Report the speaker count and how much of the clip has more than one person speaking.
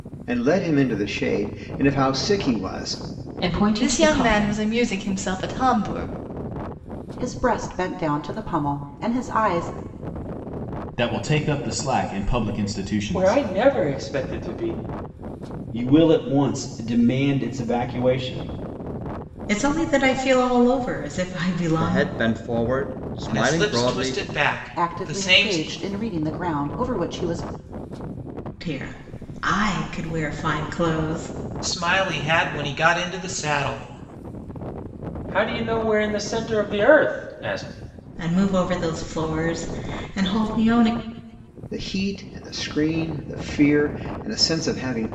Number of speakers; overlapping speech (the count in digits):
10, about 8%